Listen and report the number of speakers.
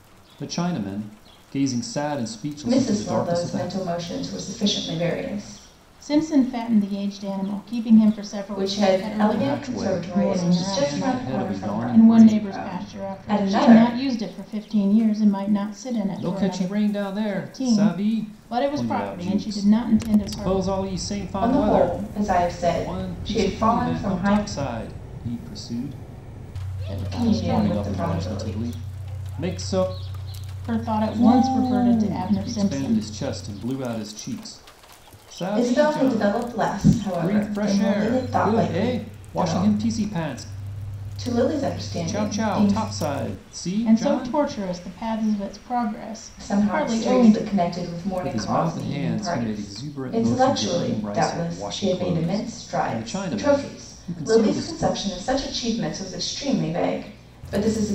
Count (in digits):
3